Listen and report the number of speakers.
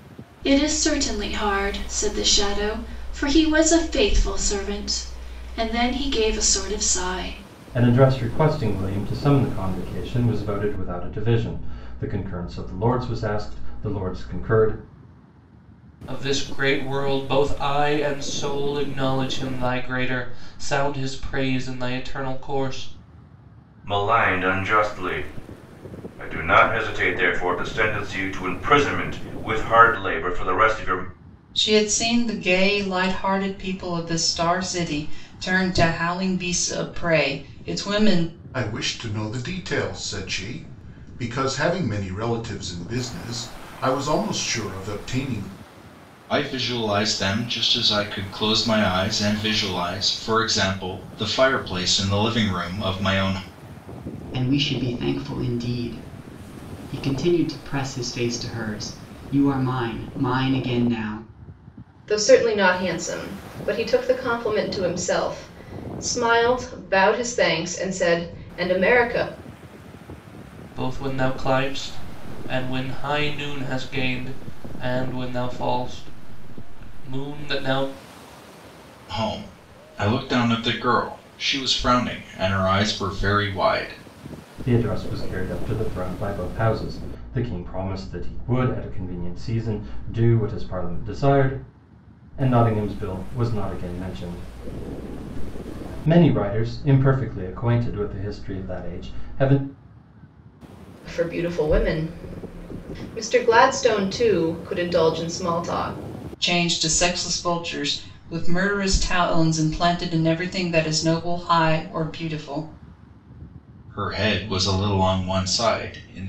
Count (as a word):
nine